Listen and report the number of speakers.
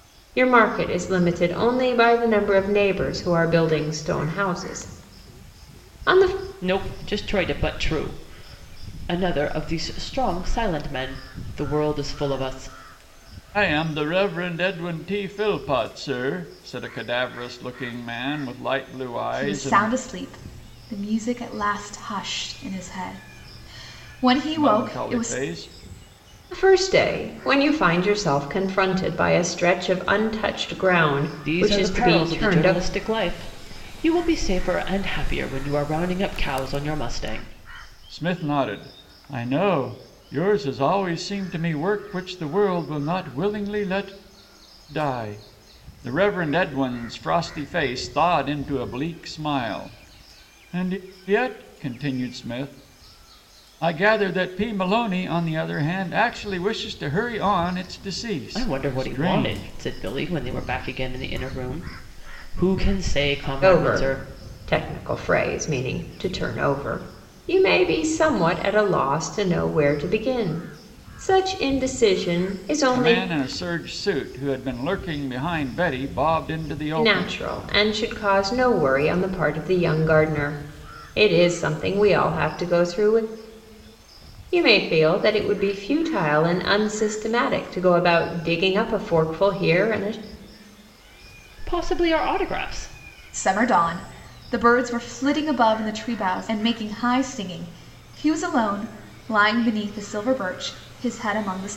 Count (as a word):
four